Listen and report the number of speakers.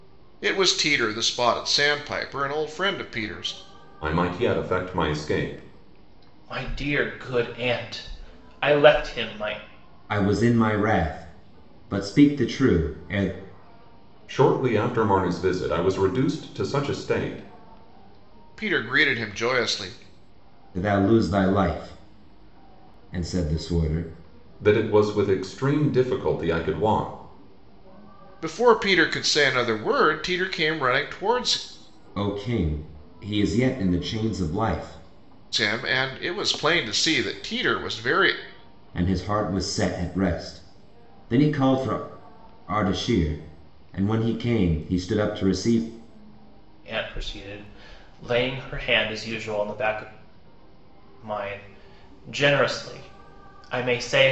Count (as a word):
four